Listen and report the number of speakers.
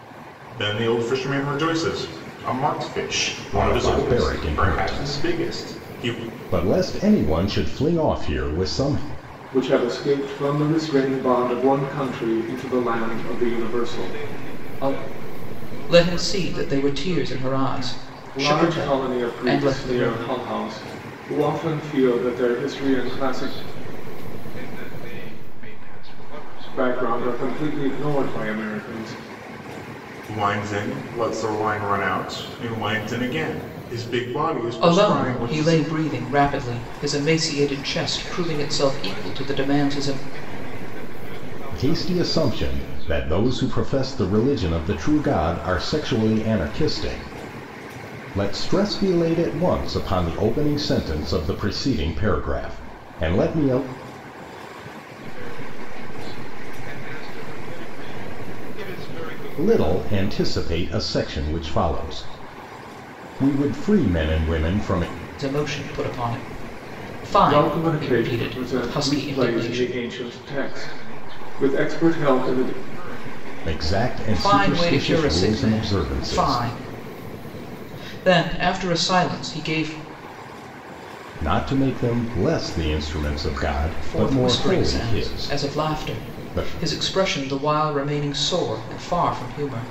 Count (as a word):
five